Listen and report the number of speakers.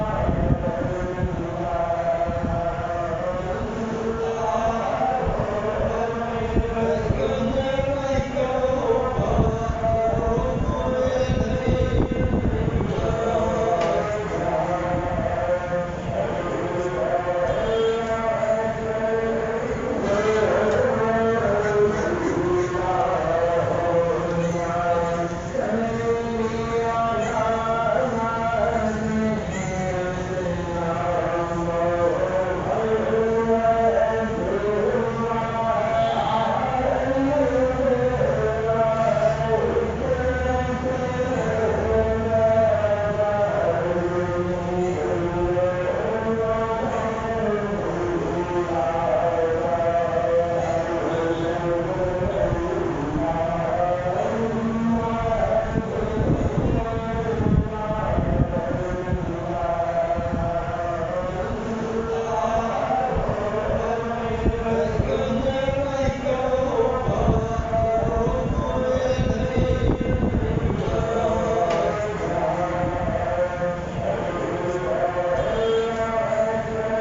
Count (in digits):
0